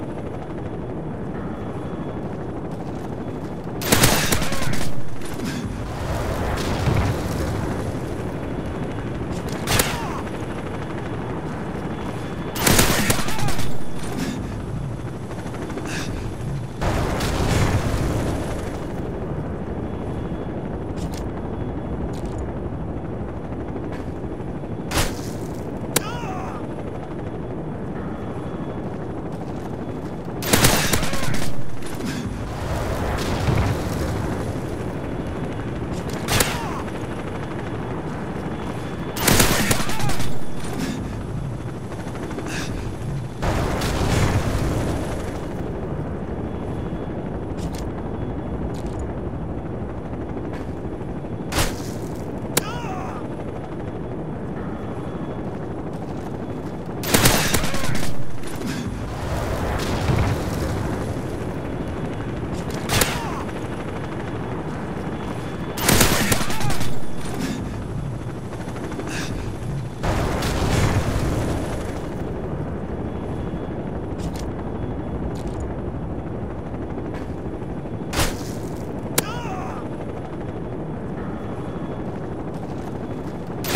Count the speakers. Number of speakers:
zero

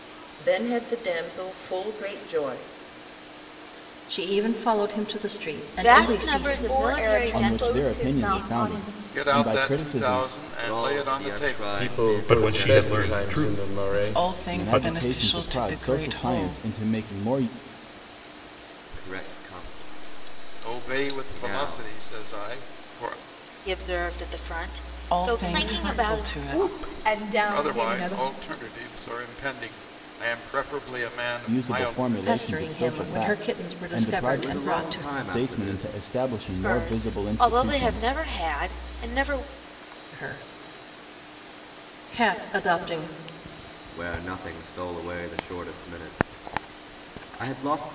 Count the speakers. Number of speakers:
ten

